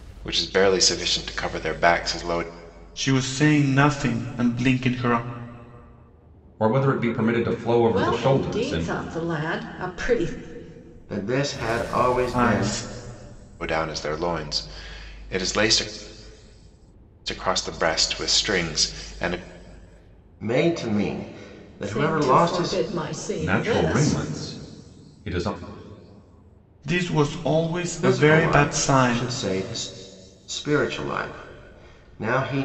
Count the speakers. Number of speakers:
five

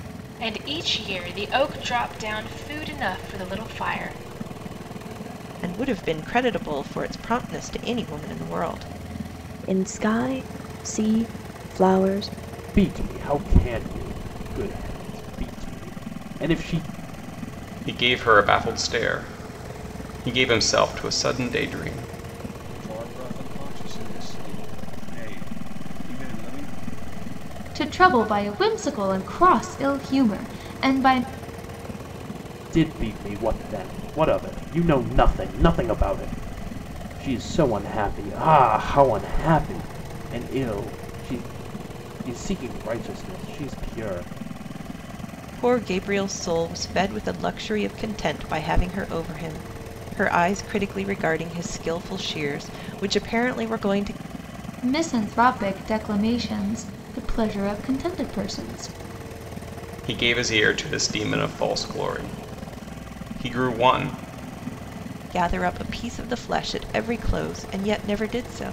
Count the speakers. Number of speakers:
seven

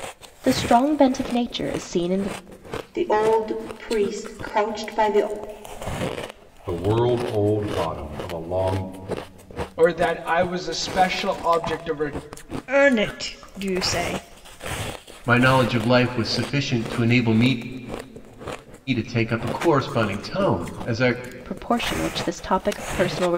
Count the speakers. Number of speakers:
six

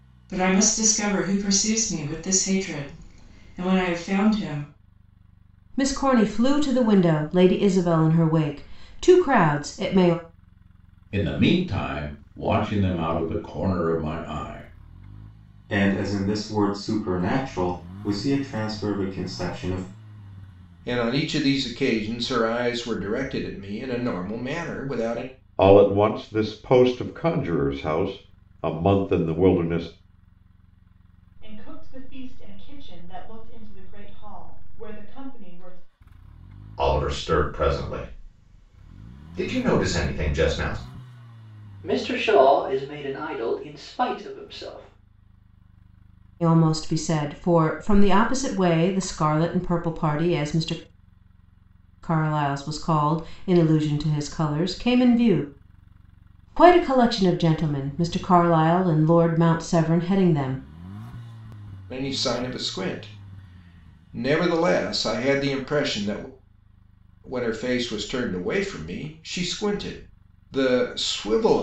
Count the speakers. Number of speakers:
nine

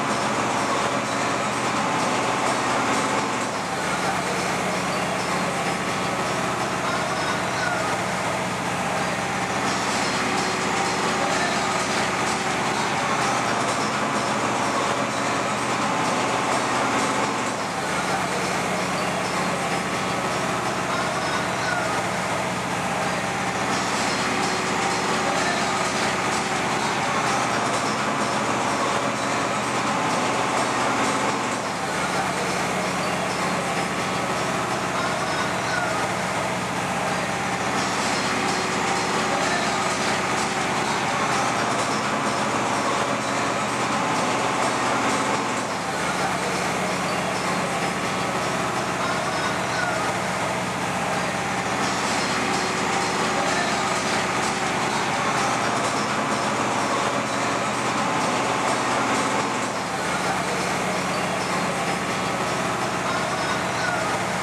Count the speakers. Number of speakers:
zero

